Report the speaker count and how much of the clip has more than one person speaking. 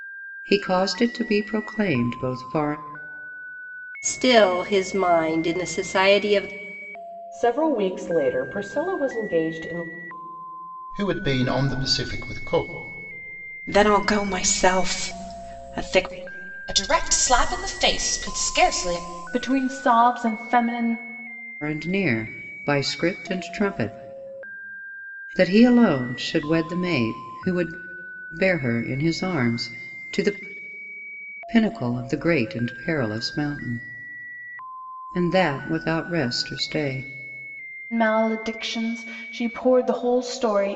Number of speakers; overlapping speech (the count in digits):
7, no overlap